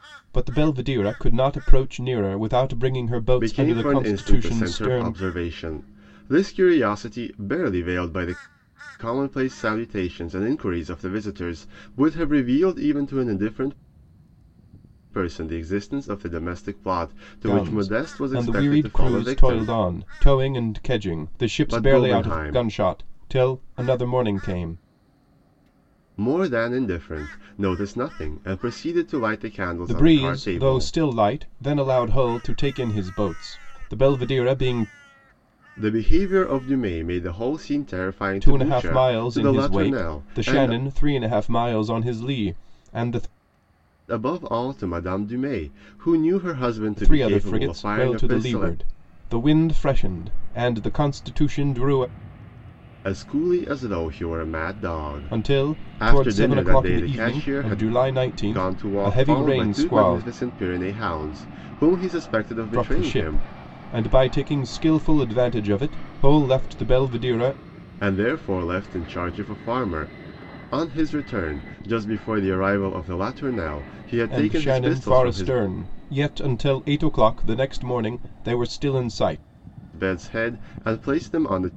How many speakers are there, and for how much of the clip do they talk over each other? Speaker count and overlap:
2, about 21%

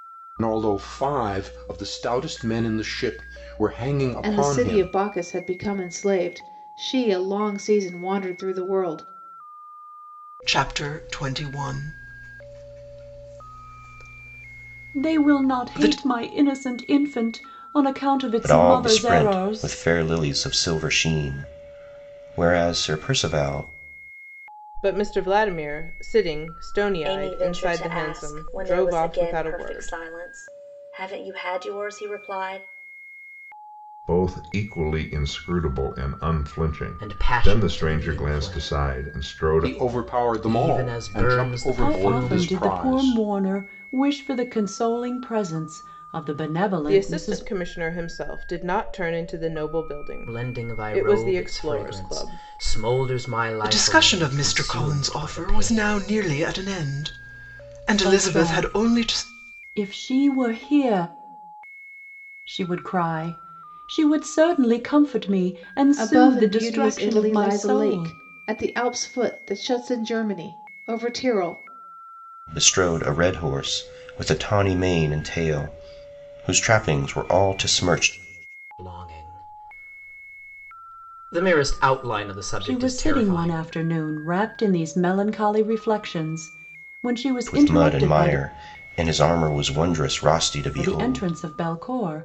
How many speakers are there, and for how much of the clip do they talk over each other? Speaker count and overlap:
9, about 26%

